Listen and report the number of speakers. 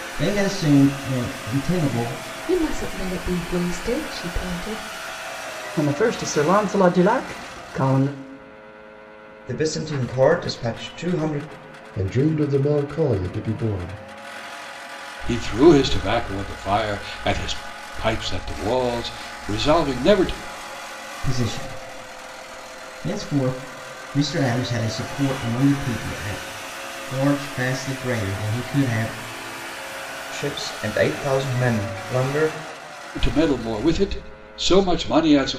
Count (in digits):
6